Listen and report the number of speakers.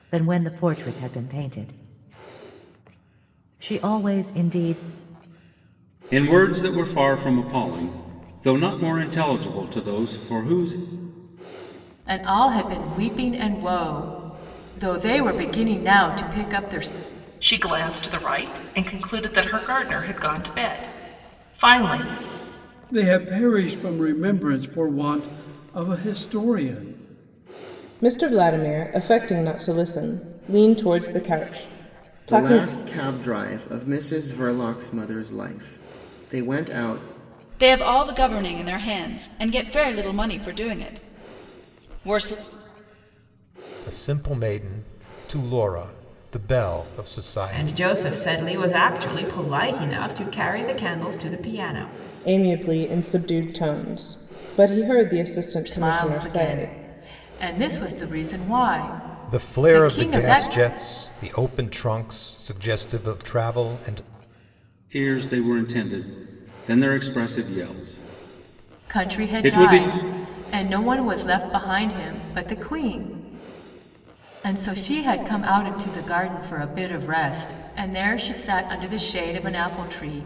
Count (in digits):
10